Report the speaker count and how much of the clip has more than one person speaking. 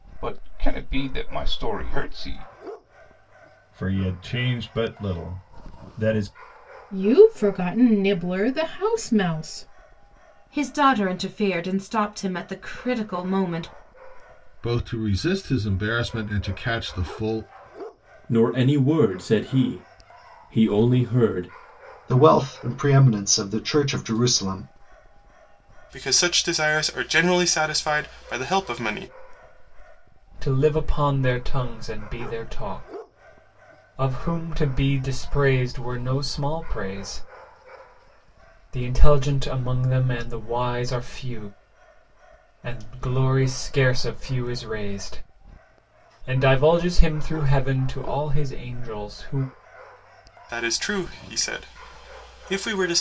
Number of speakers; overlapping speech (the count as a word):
nine, no overlap